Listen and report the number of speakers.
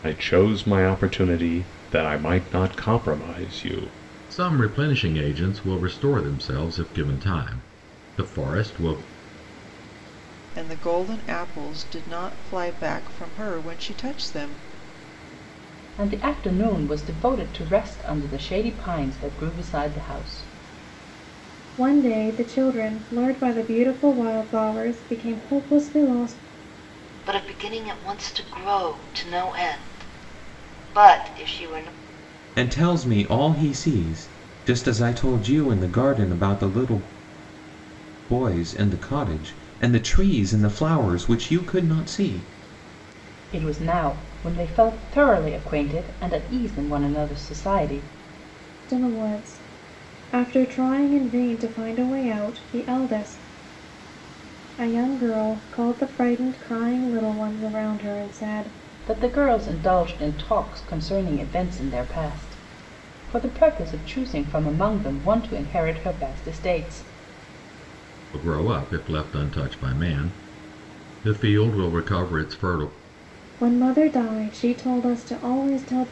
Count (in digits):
7